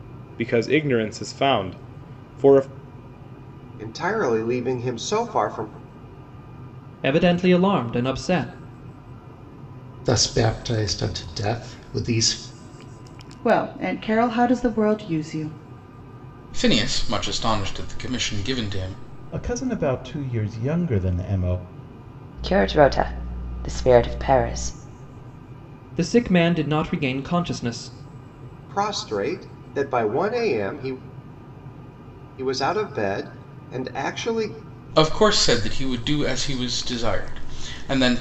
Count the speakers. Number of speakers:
8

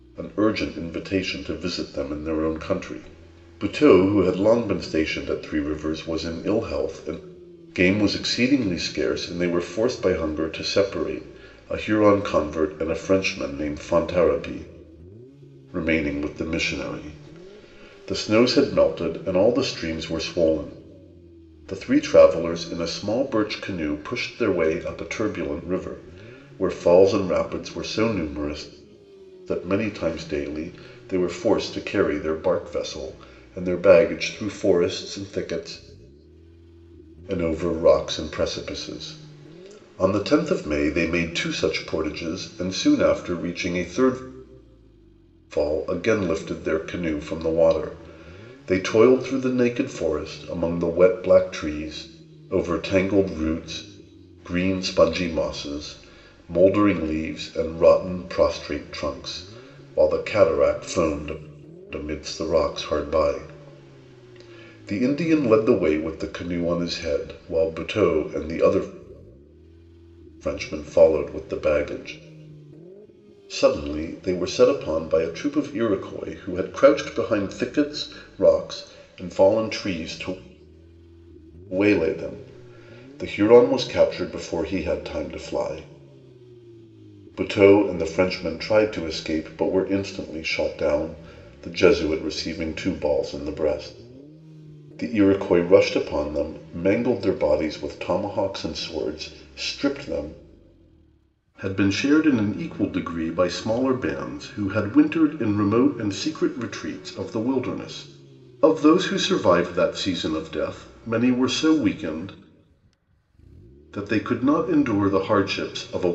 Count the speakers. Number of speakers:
1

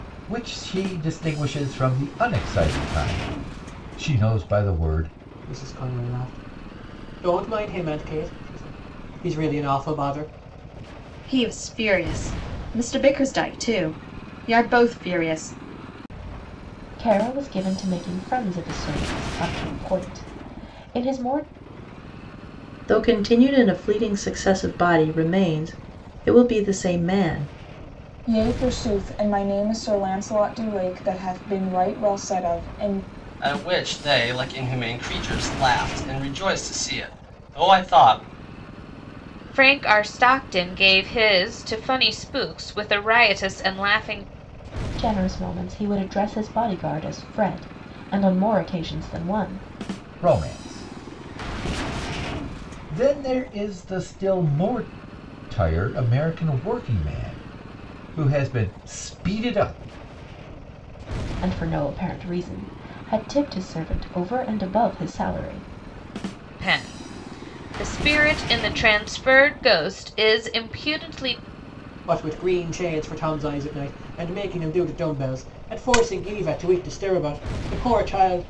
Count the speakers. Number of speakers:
8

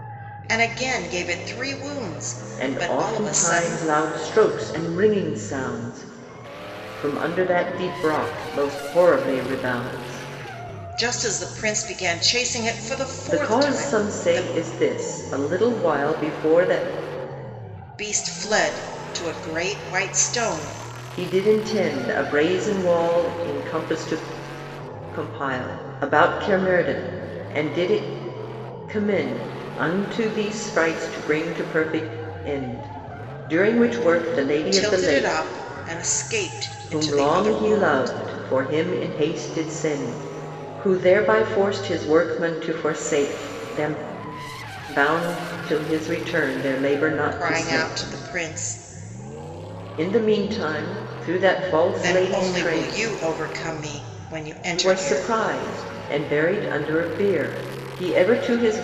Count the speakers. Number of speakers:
2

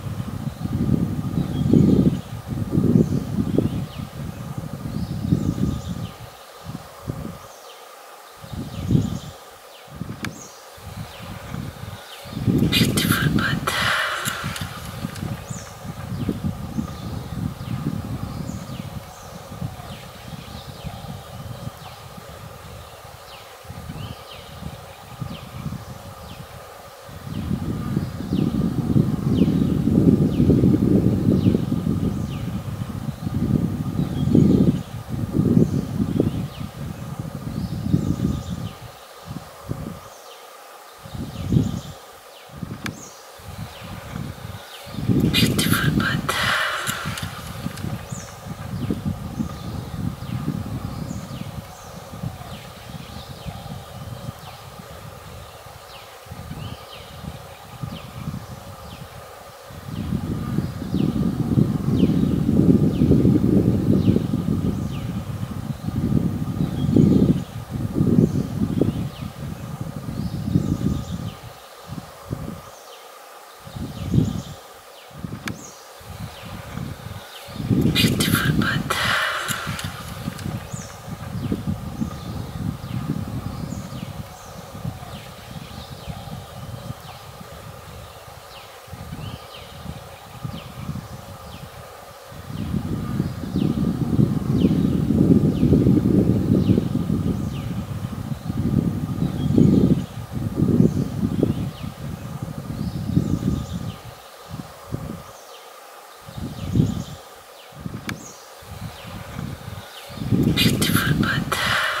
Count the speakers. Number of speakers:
0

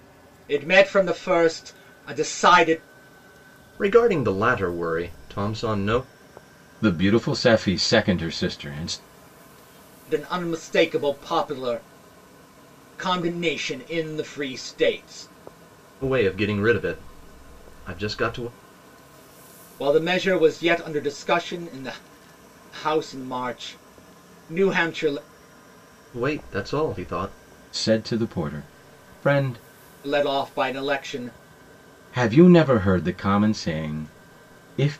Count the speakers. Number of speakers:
3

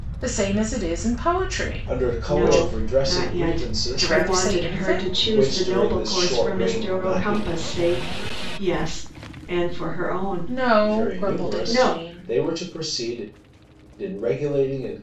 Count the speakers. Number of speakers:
3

